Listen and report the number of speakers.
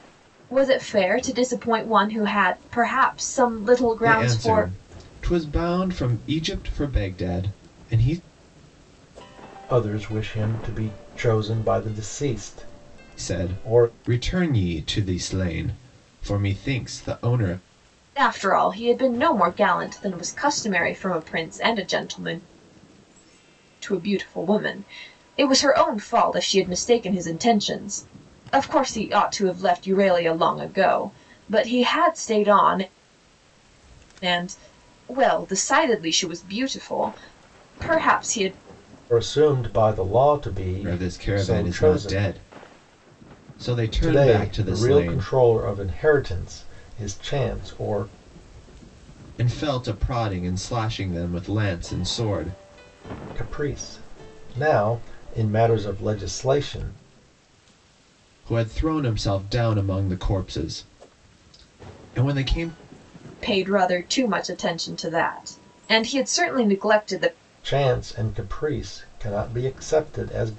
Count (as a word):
three